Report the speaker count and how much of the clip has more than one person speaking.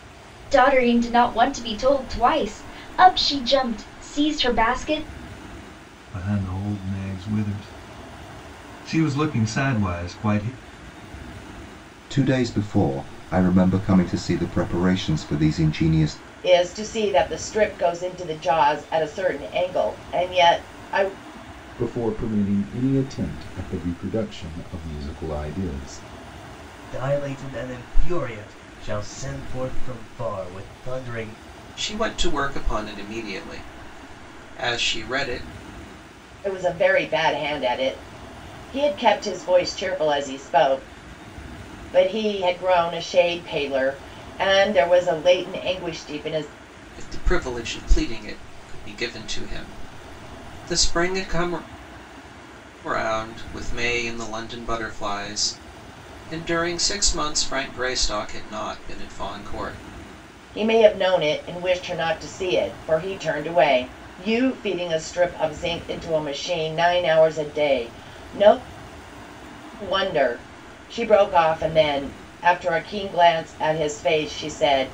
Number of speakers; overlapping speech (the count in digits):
7, no overlap